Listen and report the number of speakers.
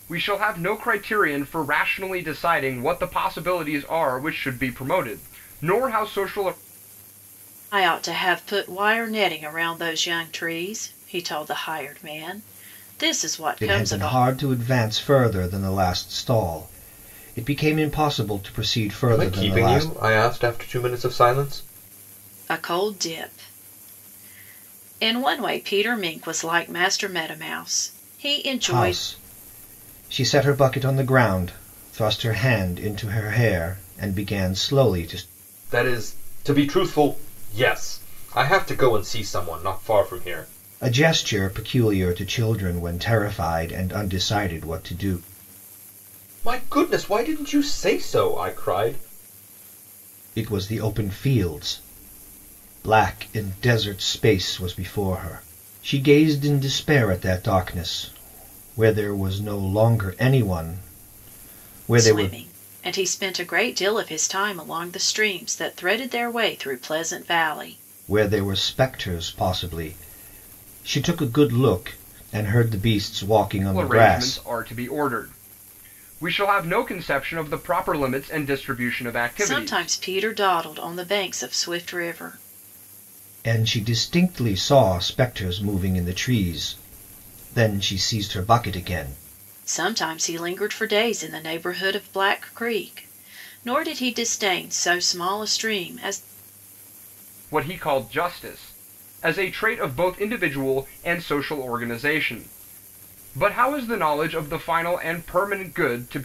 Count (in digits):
4